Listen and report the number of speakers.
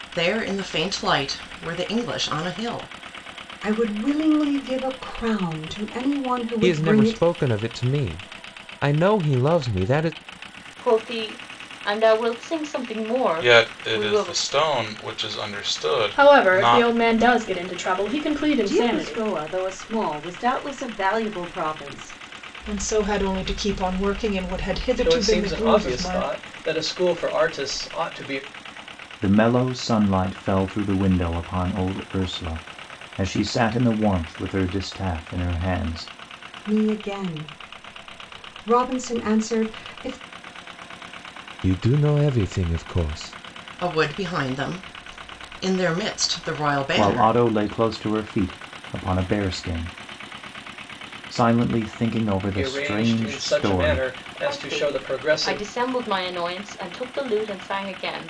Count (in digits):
10